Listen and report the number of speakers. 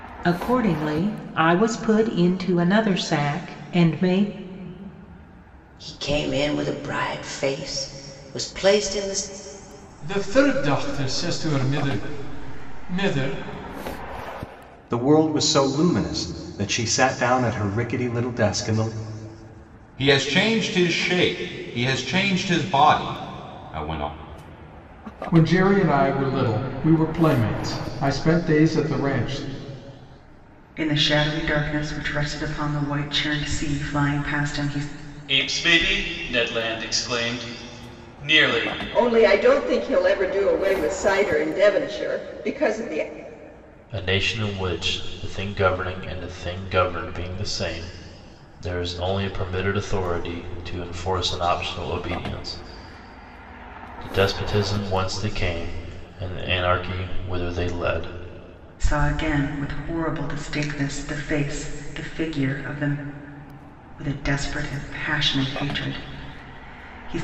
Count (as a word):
ten